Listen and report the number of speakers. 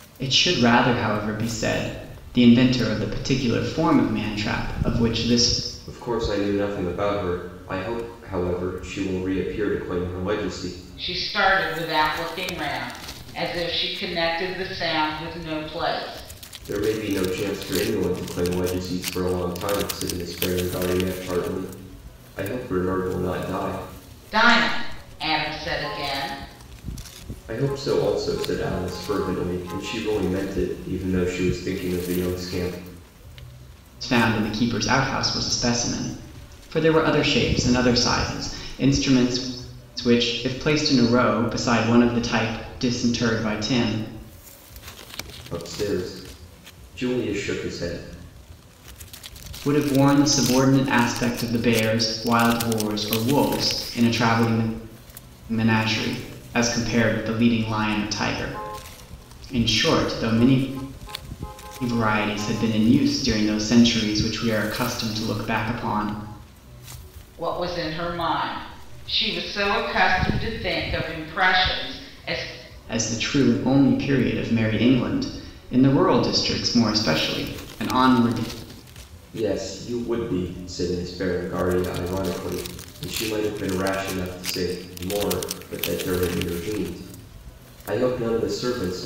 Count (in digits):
3